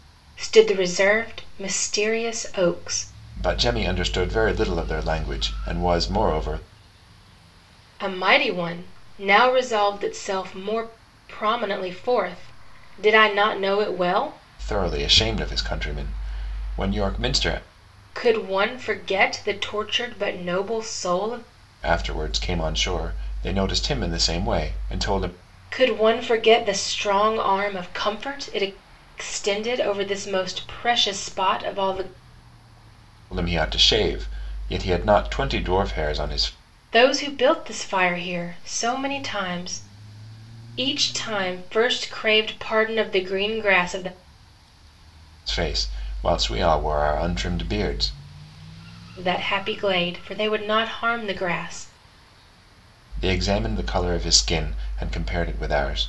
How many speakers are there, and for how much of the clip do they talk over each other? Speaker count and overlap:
2, no overlap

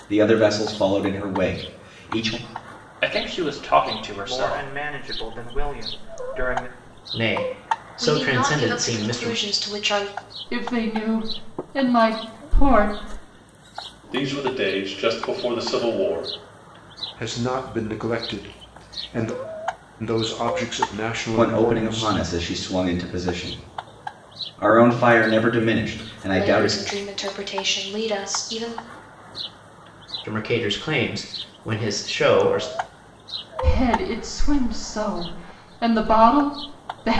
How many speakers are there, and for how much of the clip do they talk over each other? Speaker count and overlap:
8, about 9%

